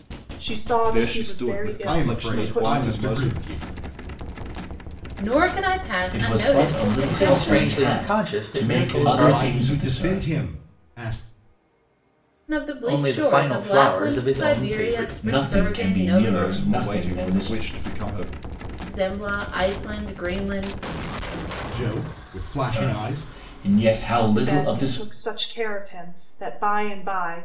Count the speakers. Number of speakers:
6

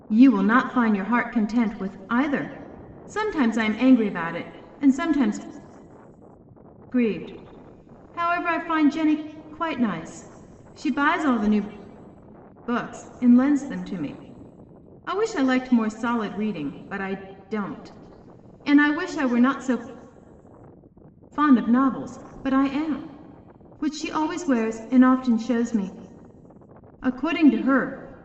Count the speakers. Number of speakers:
1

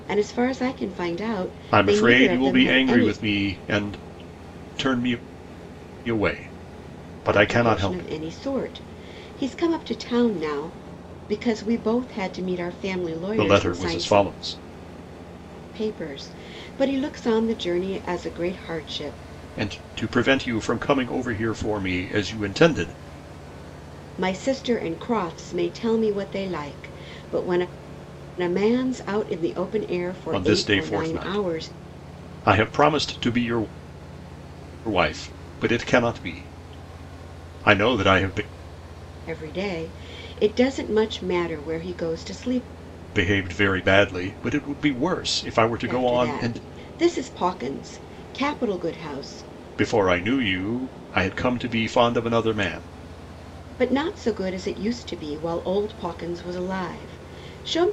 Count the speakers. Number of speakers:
2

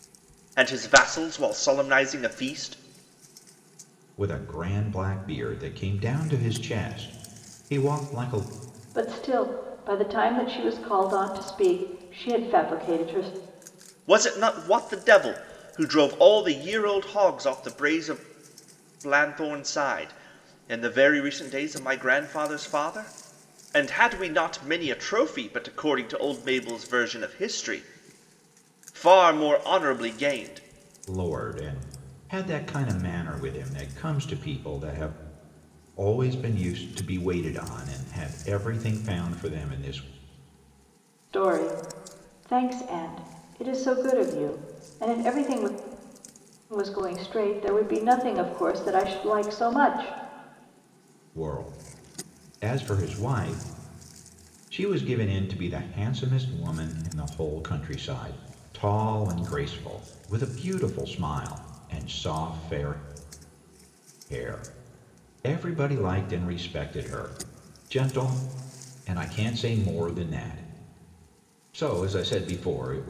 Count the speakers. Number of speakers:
3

